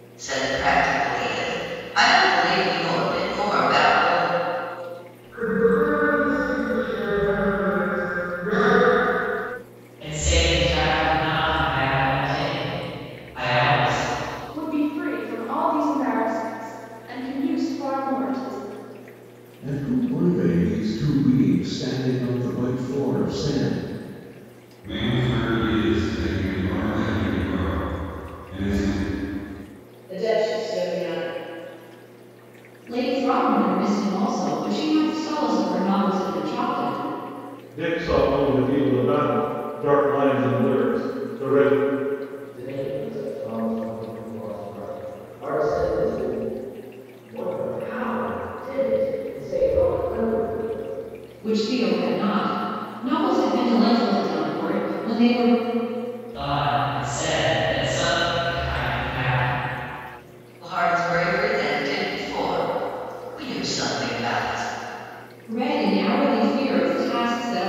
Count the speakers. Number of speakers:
10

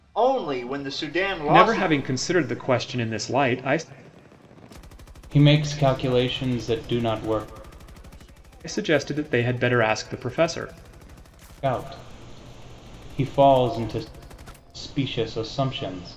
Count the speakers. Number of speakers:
3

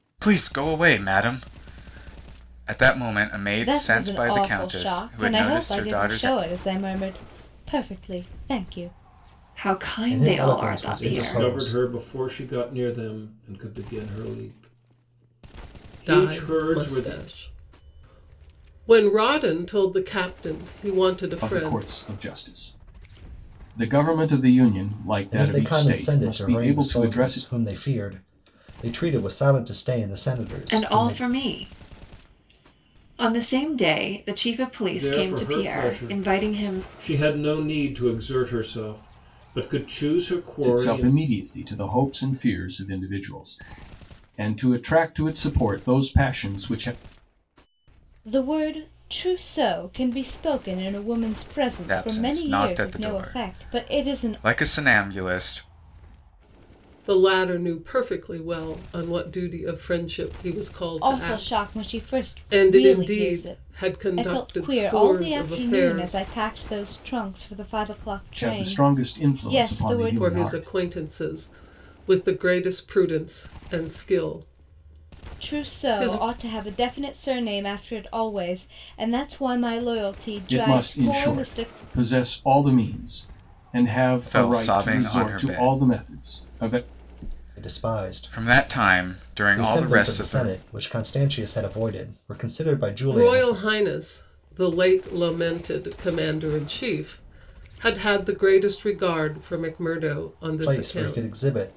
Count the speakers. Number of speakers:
7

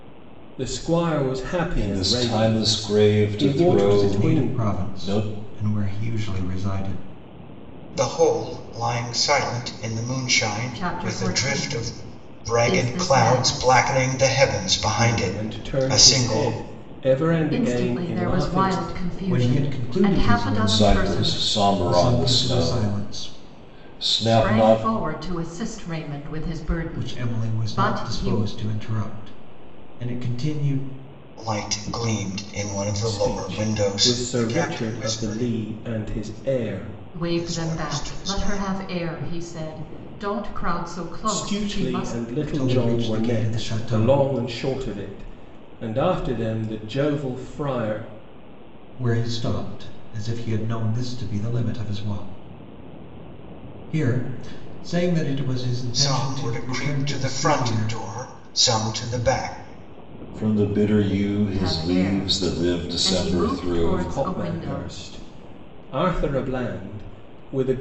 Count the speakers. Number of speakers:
5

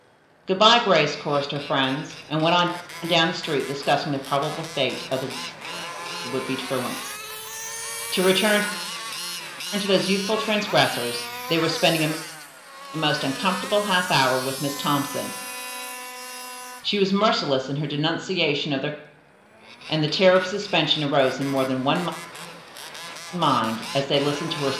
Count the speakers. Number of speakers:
1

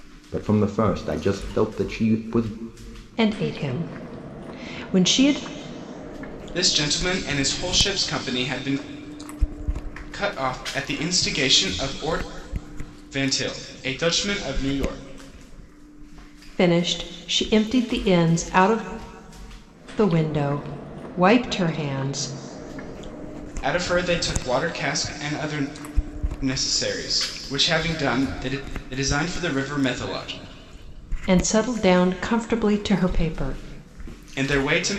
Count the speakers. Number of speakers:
3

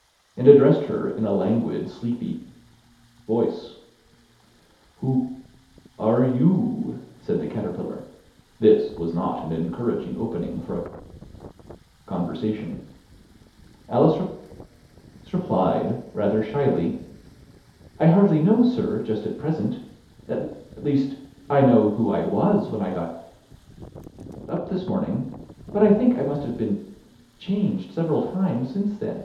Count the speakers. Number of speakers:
1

